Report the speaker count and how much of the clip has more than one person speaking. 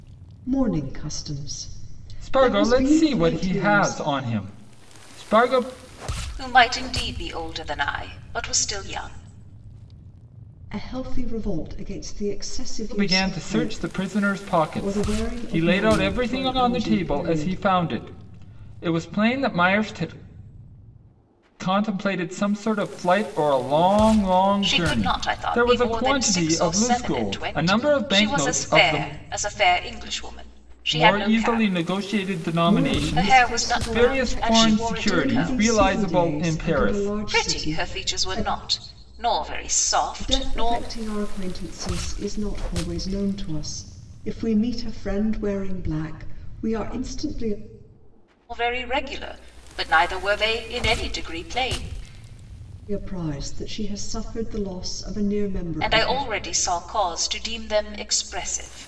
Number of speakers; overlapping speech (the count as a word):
three, about 29%